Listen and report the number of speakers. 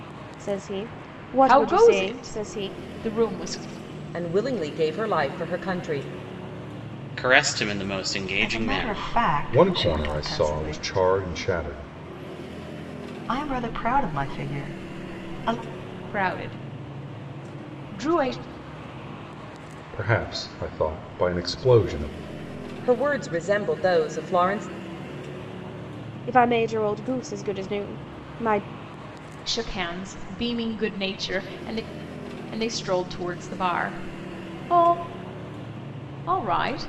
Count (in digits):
6